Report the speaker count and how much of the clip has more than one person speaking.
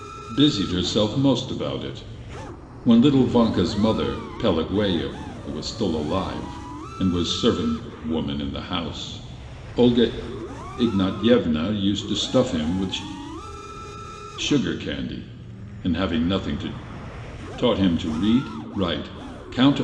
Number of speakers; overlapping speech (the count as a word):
one, no overlap